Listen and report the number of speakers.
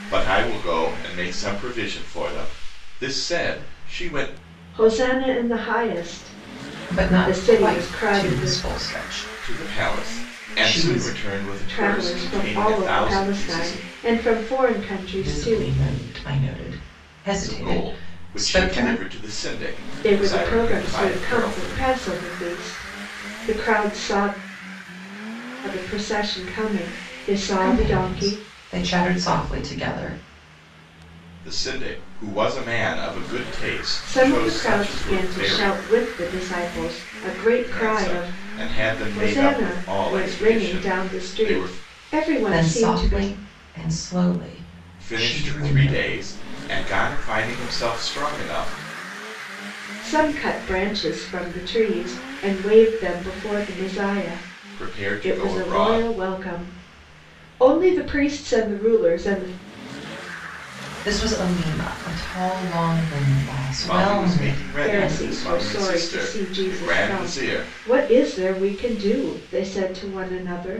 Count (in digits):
3